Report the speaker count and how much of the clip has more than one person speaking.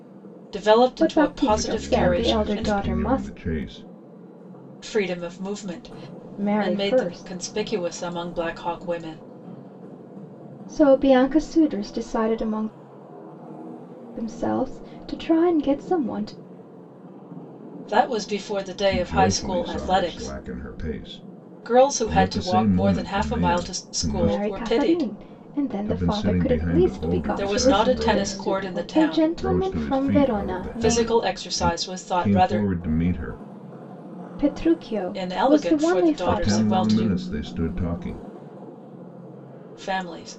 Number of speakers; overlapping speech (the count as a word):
three, about 41%